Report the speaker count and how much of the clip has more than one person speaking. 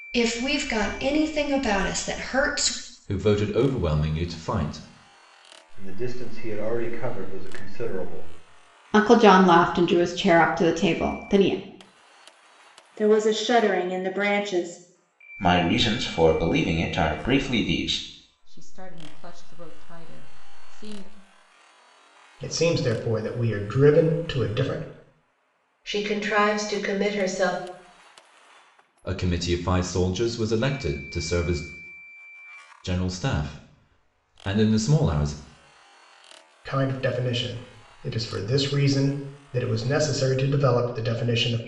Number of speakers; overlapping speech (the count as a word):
nine, no overlap